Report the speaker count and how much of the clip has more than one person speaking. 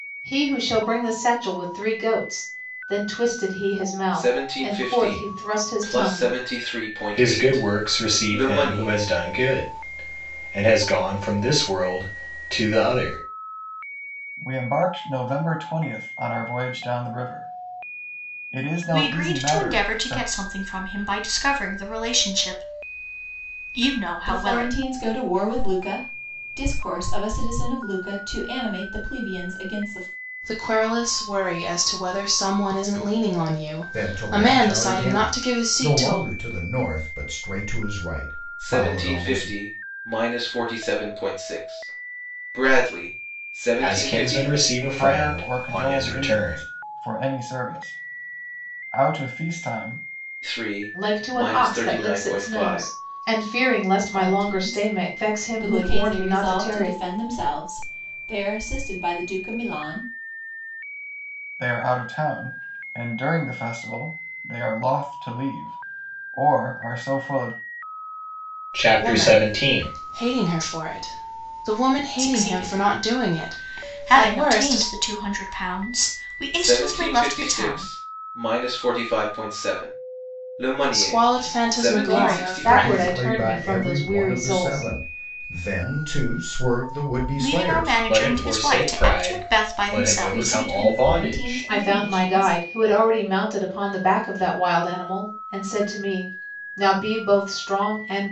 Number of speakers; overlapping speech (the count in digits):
8, about 32%